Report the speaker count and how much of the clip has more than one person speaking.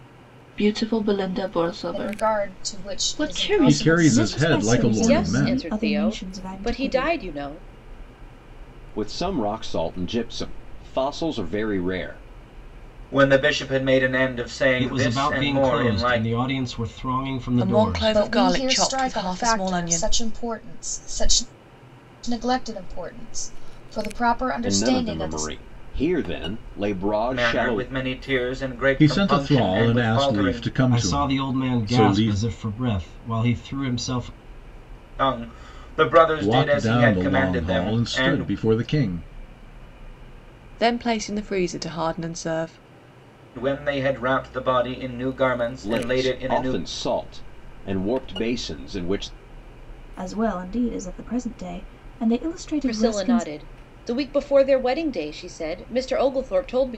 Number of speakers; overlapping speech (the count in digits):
9, about 32%